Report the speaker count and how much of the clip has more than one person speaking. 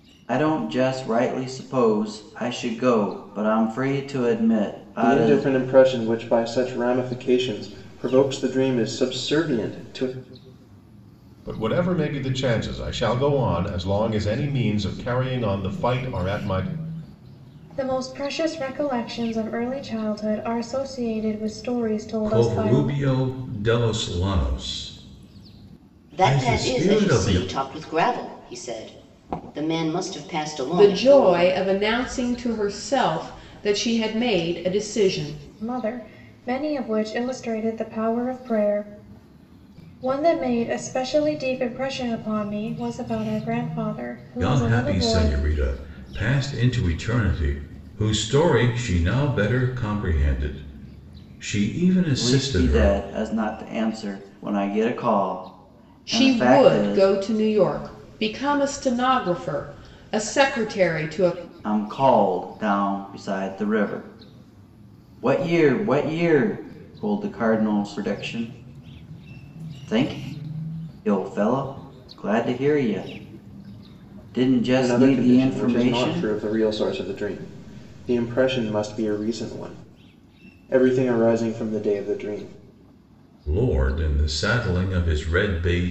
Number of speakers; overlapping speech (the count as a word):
seven, about 9%